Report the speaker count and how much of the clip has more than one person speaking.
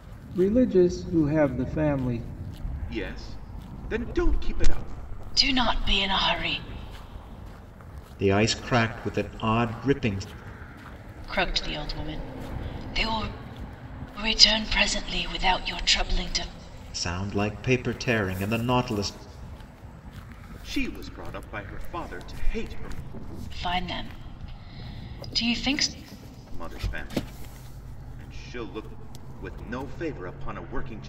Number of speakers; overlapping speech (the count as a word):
four, no overlap